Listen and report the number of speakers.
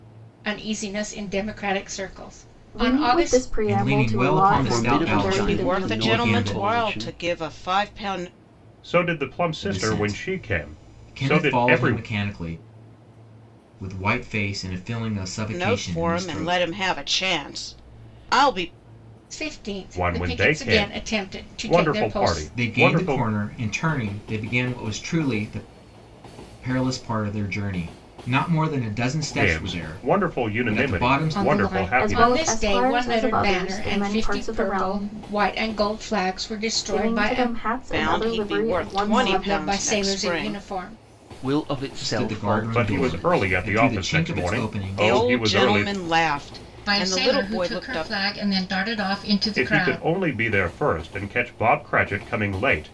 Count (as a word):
six